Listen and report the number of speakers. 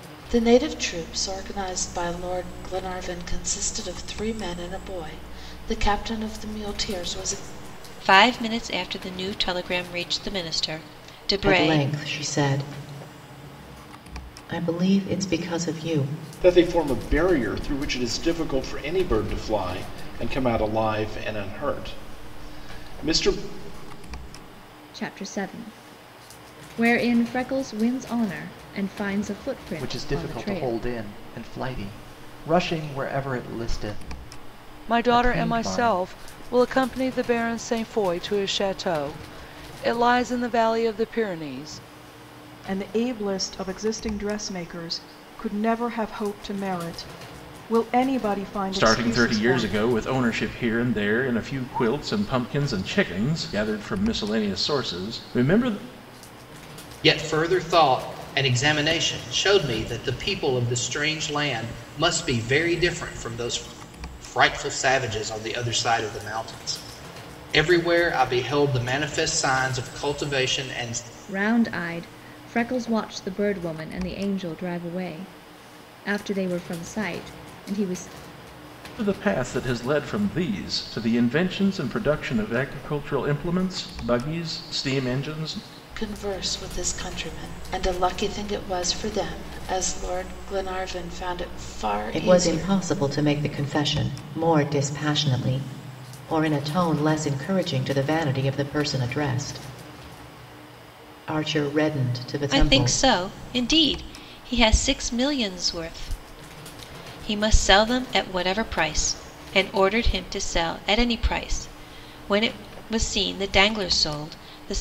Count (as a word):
ten